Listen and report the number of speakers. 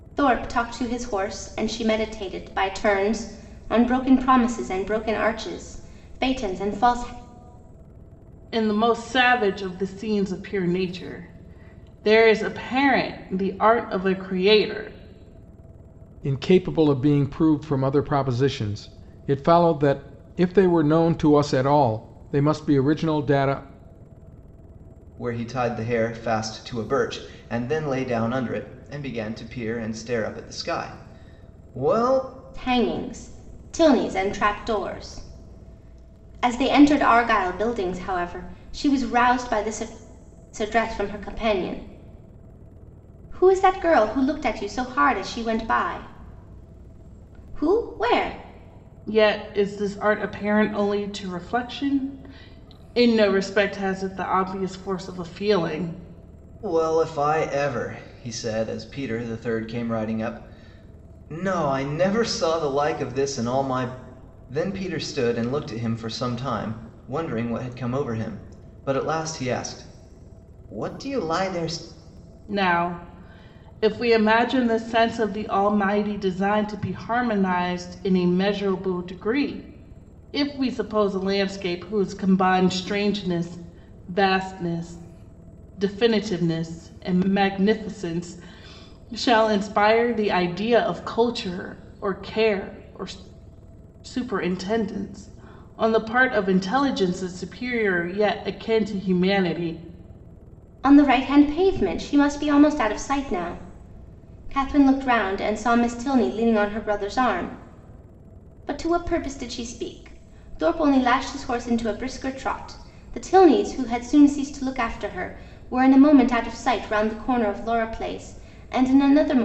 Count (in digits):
4